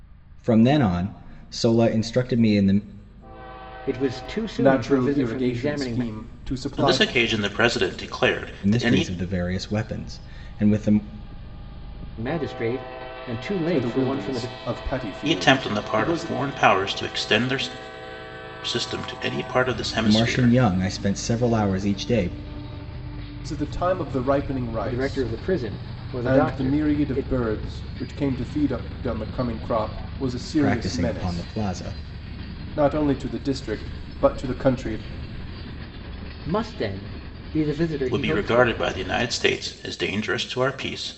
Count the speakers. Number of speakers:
4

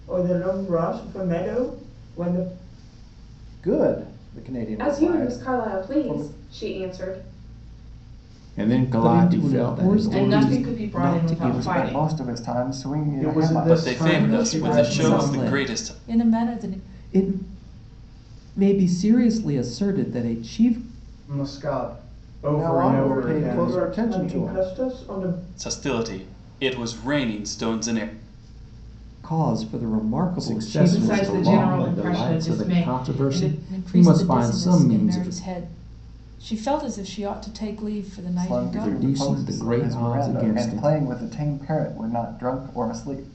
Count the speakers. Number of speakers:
10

